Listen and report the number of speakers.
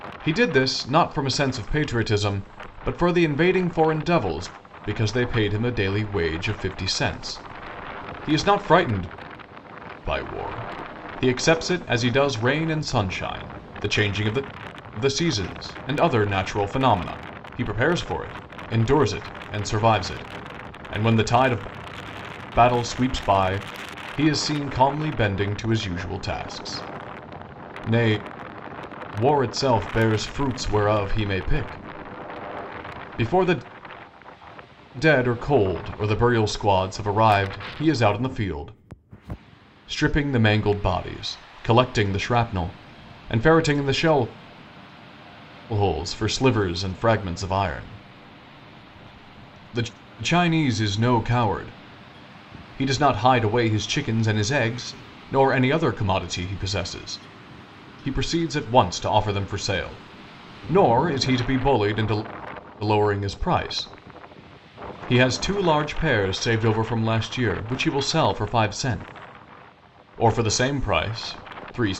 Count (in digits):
1